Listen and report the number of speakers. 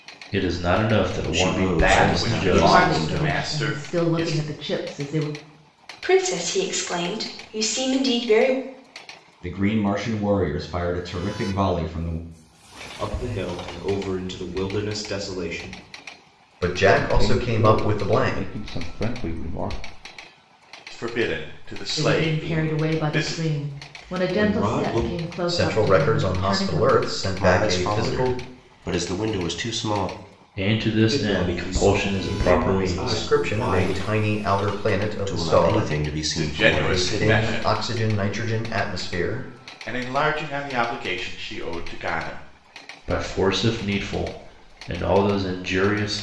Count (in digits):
9